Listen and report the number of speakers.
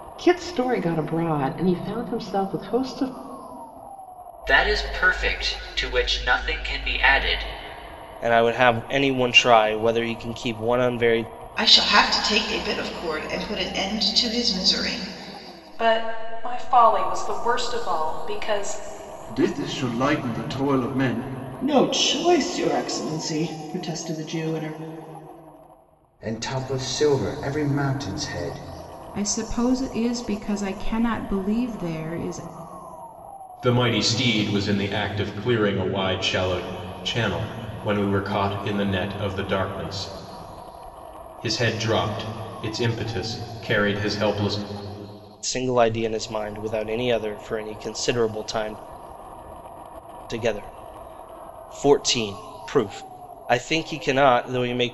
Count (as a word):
ten